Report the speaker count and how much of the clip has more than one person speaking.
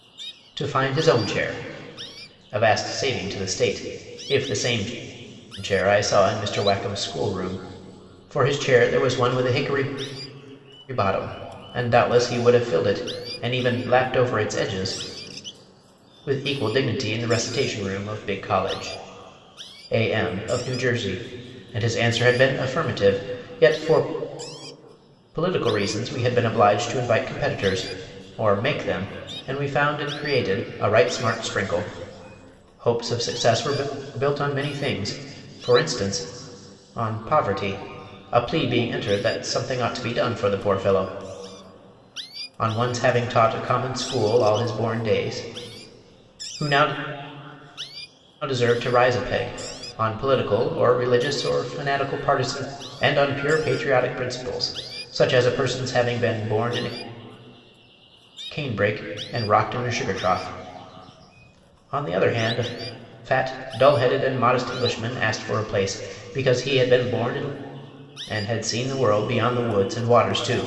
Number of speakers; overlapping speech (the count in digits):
1, no overlap